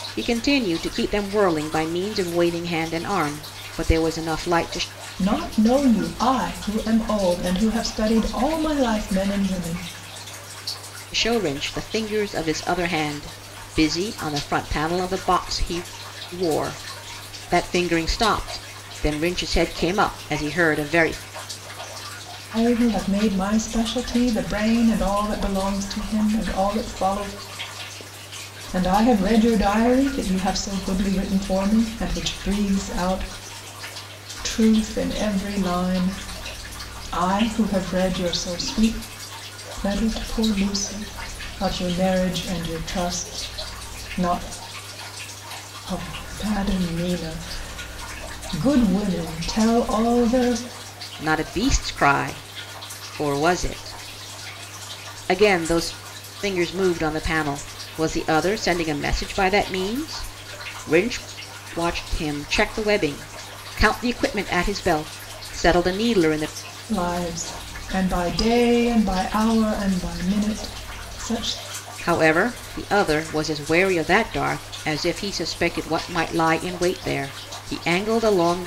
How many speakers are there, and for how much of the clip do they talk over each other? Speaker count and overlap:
2, no overlap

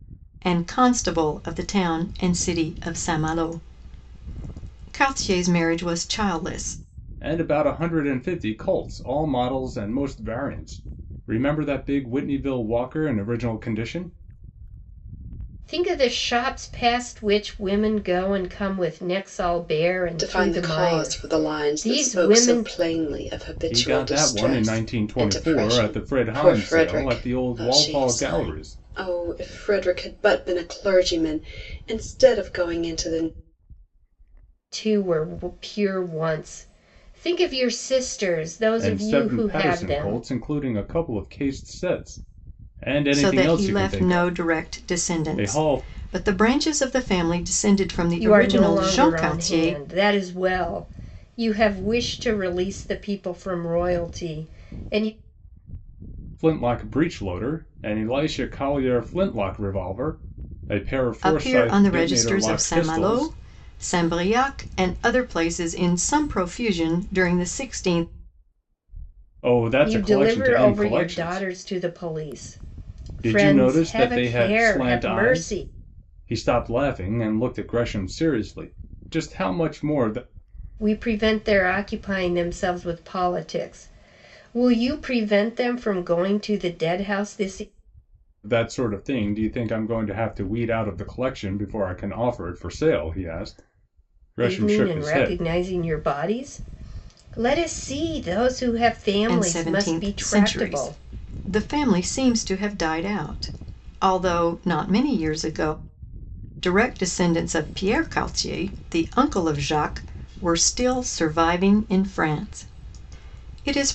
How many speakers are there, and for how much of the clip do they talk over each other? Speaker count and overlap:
4, about 20%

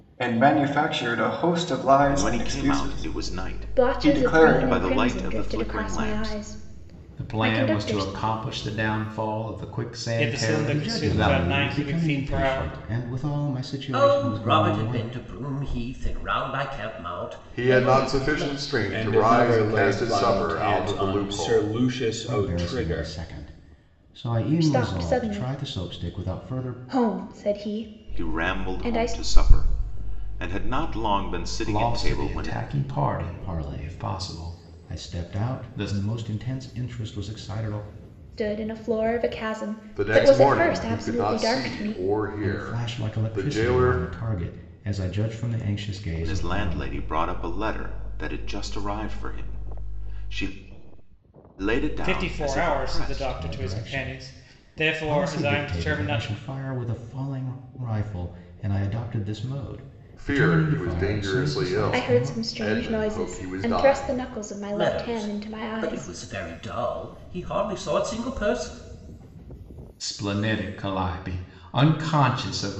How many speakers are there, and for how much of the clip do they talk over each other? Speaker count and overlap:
9, about 48%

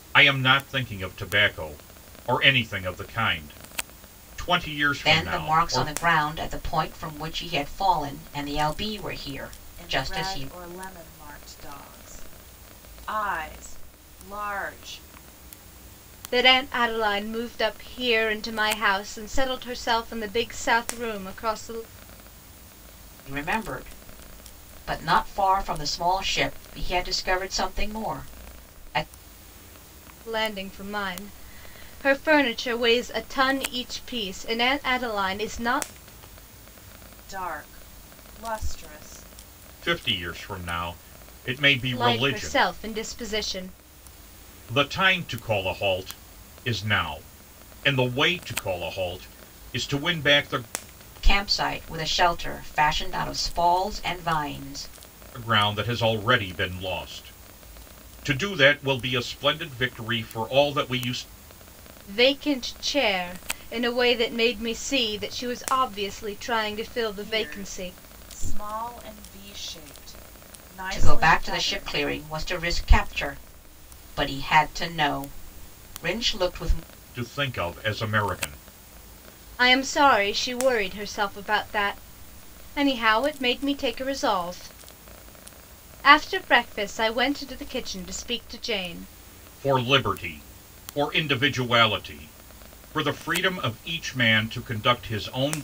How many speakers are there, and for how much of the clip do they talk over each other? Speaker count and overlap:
4, about 5%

